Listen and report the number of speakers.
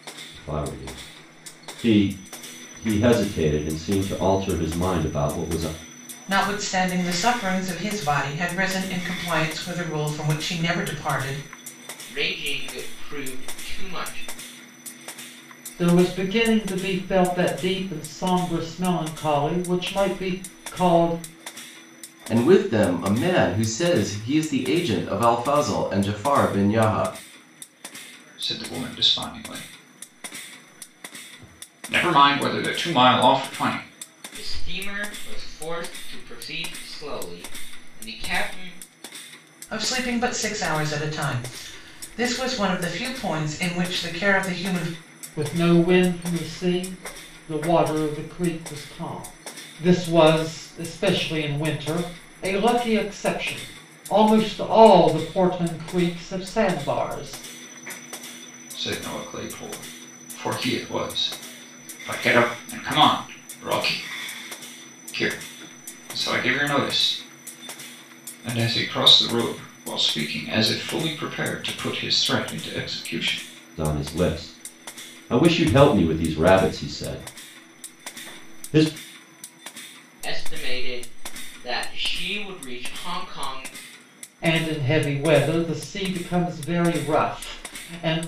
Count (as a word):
six